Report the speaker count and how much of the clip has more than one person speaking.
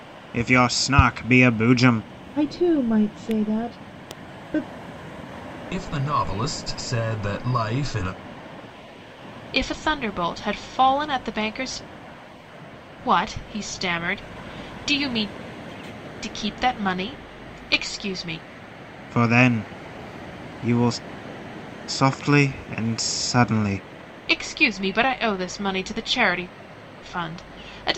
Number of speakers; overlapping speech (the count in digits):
4, no overlap